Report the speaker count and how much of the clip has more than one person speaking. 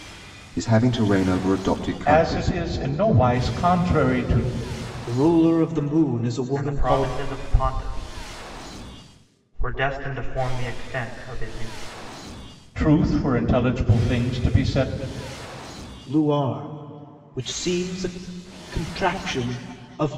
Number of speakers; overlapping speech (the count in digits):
4, about 6%